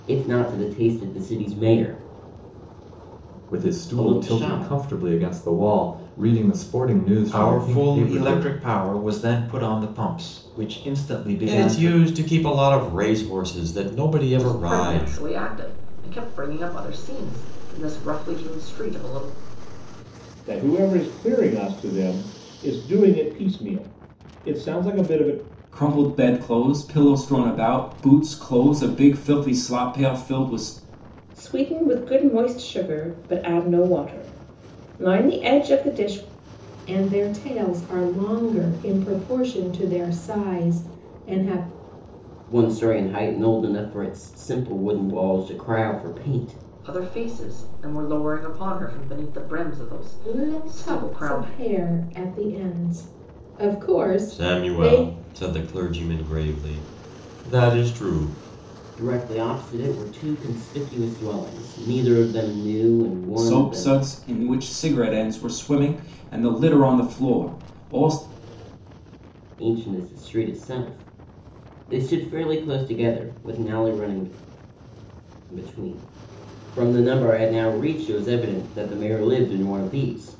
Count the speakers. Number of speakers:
9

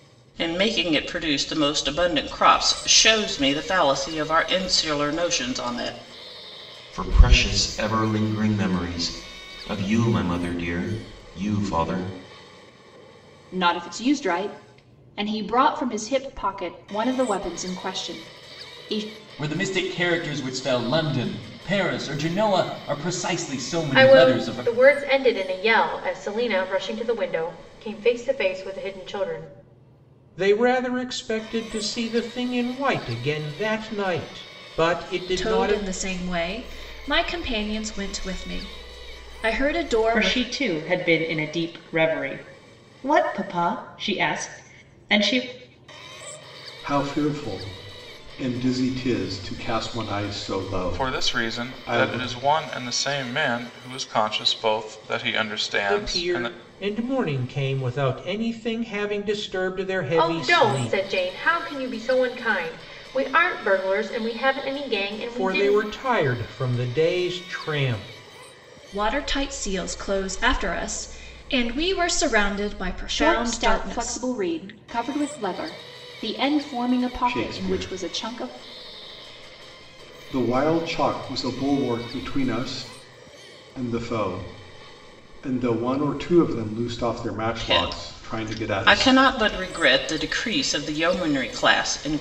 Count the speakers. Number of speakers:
10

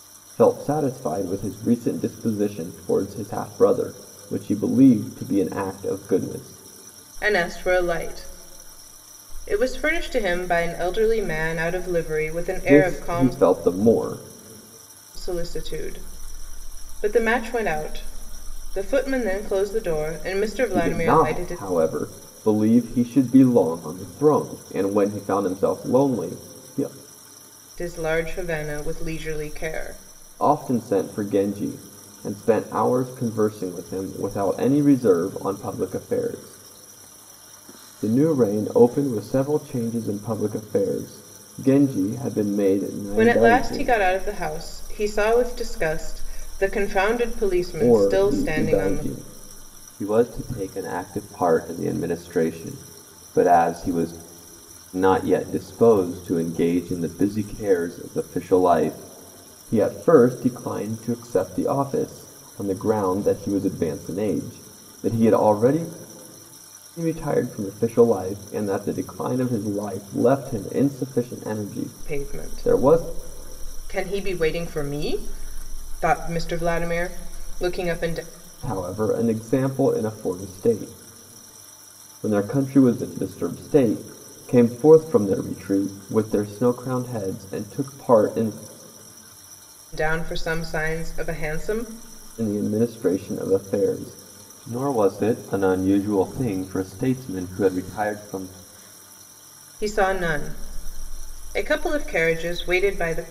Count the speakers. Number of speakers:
2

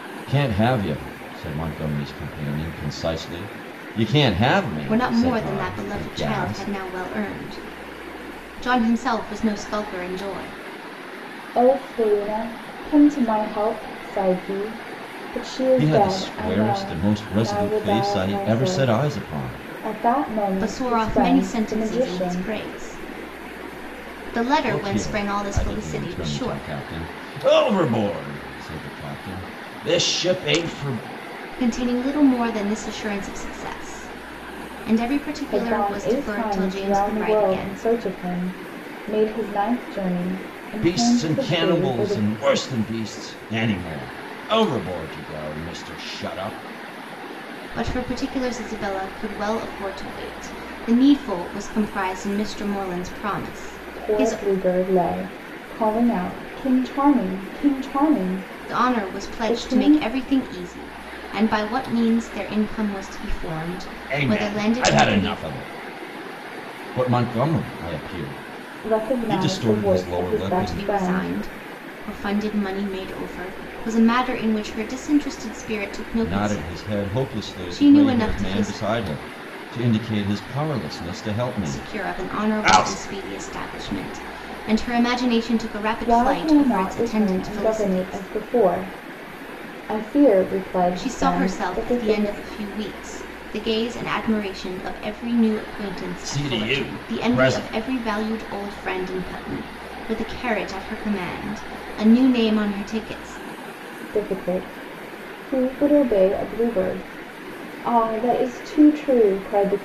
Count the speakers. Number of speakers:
3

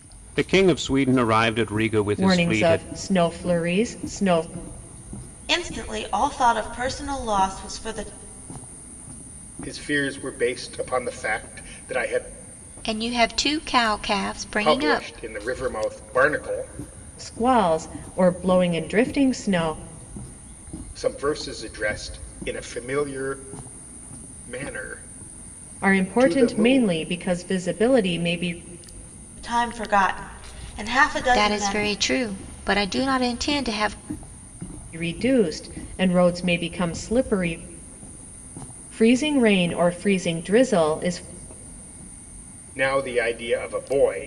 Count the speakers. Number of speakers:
5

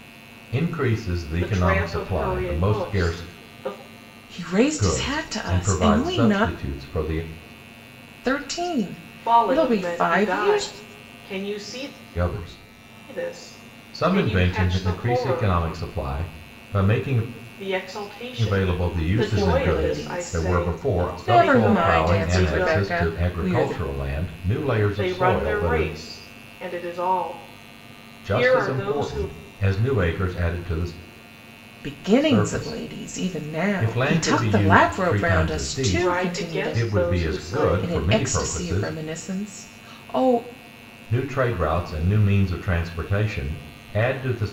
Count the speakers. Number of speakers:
3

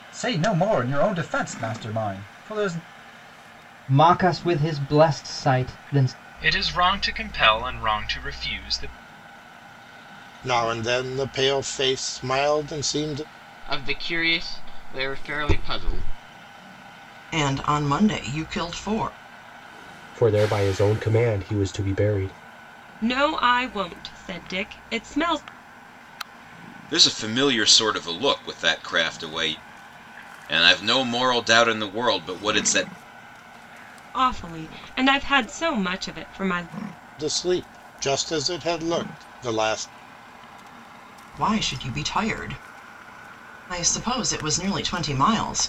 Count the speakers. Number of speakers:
9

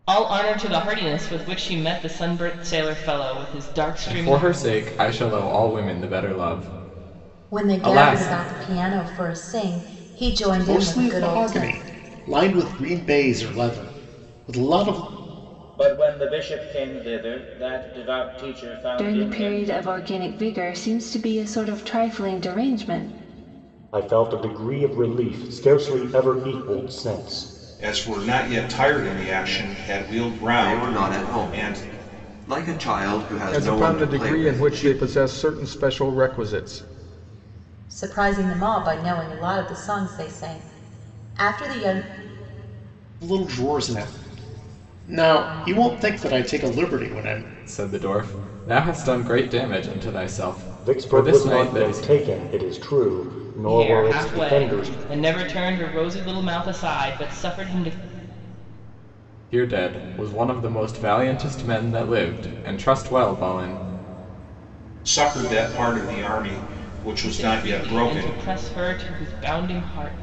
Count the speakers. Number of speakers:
10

